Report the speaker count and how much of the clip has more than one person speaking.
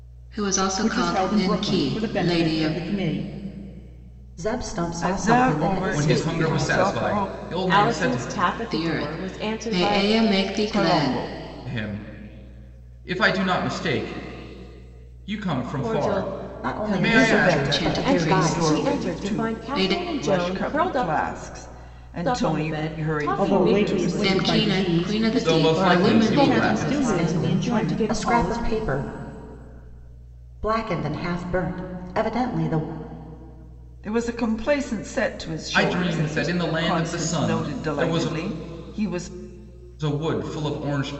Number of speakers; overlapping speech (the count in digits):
6, about 50%